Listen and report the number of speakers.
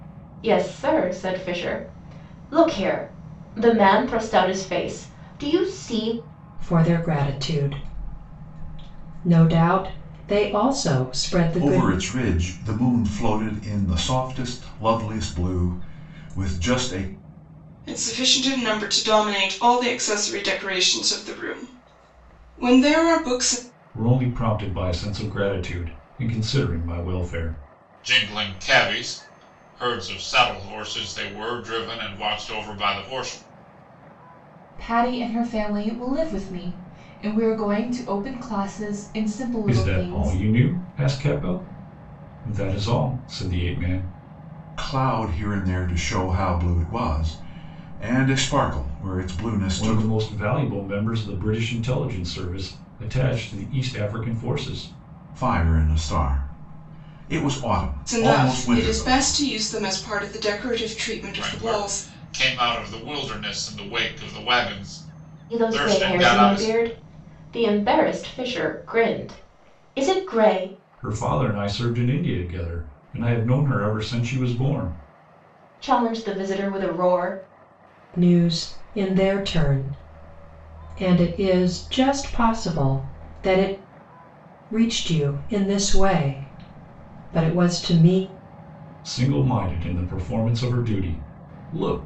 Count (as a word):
seven